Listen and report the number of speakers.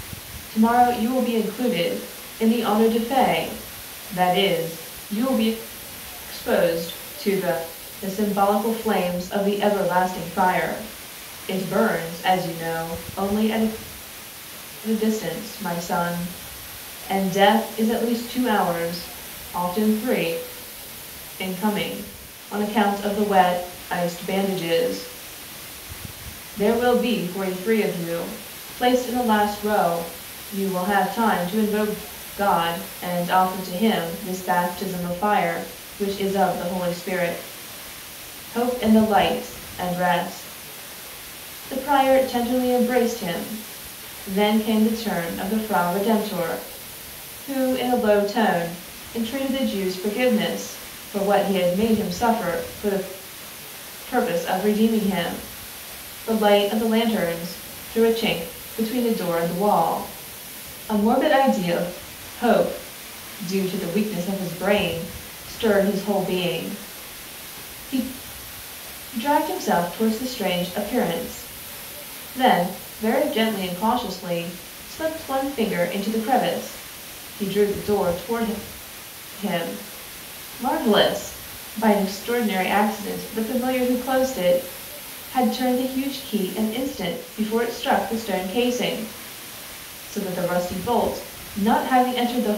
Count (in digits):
1